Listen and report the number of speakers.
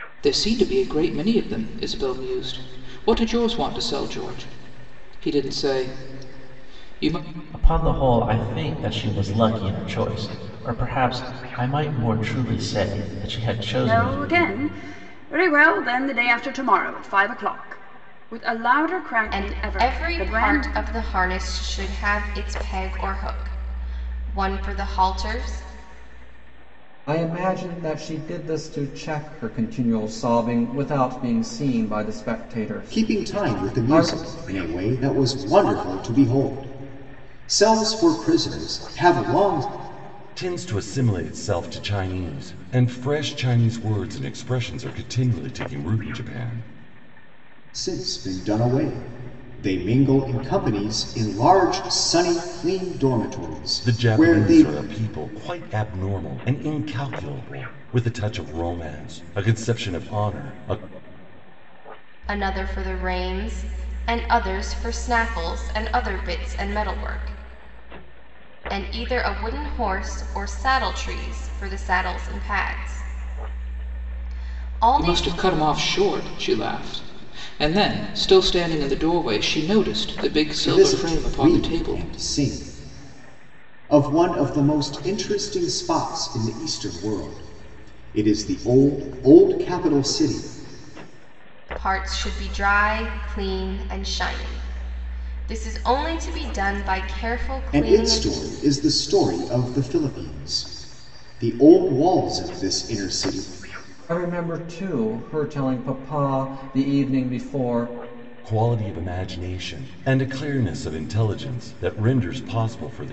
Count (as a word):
seven